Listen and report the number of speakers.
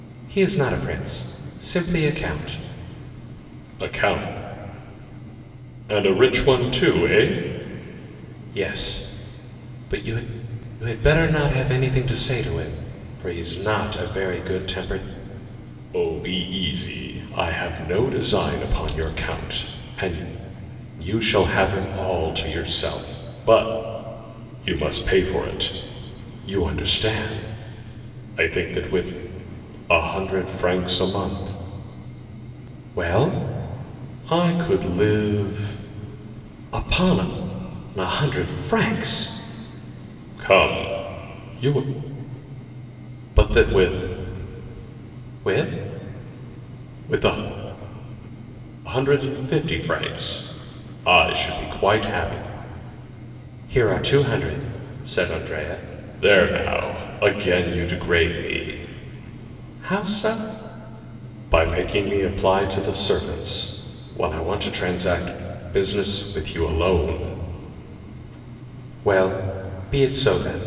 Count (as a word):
one